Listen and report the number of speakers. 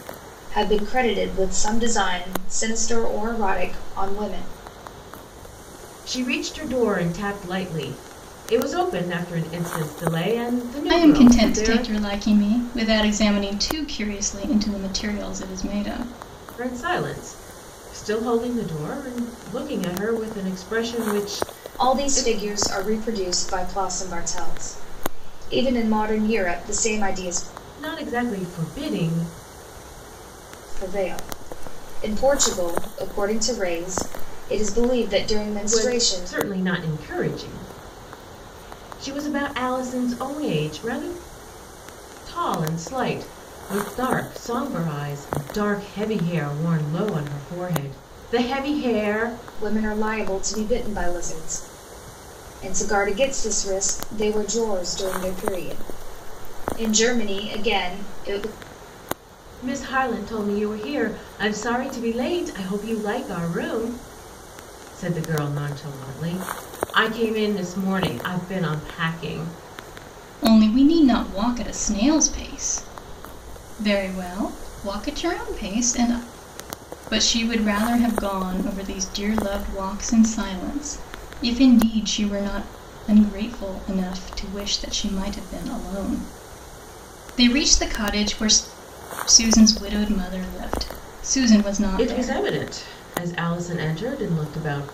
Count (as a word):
three